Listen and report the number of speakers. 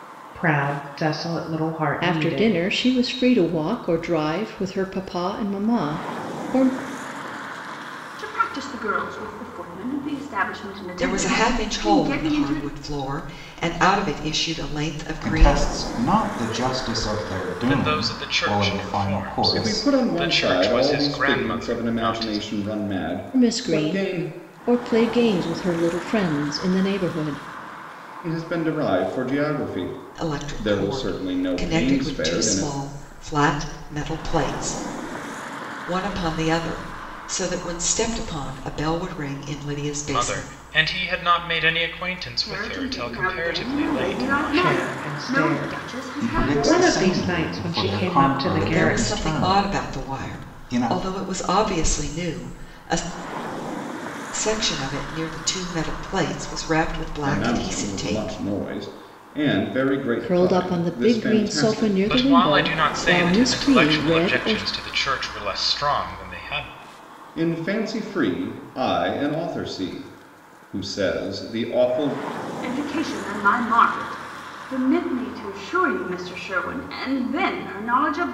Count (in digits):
7